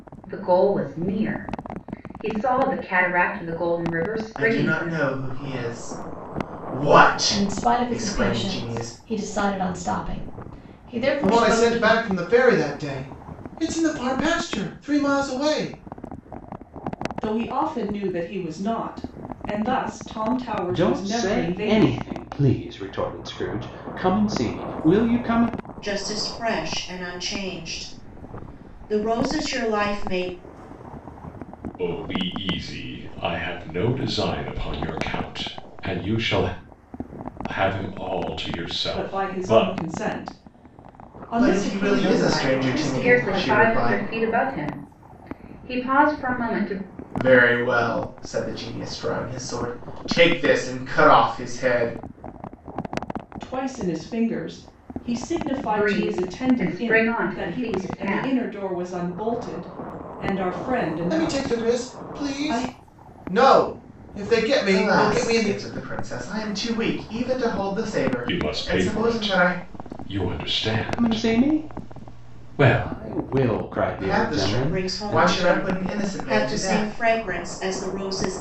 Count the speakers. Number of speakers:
8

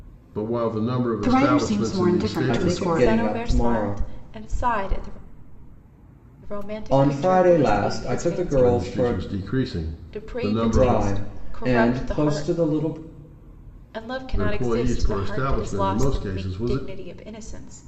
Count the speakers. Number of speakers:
4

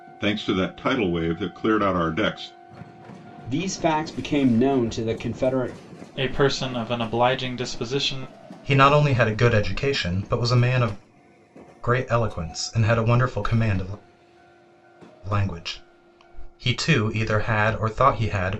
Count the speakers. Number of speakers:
4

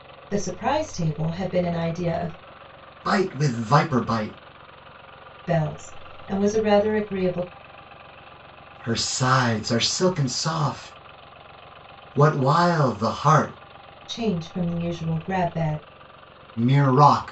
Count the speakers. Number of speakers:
2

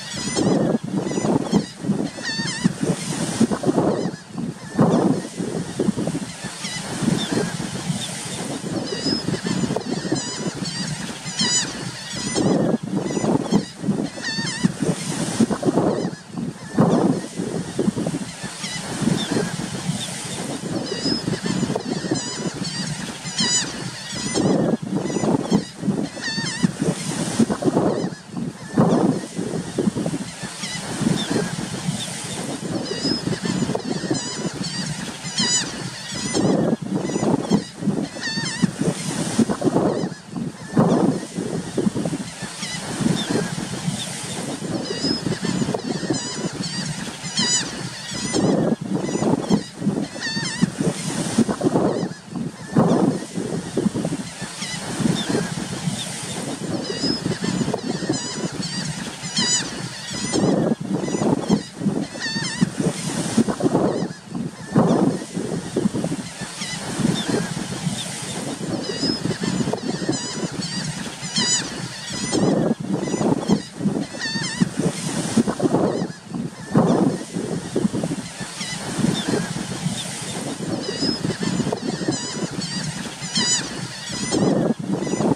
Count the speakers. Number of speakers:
0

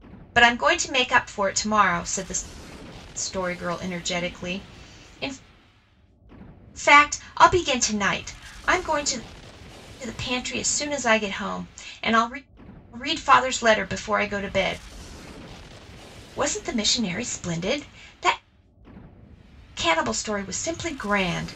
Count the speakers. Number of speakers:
1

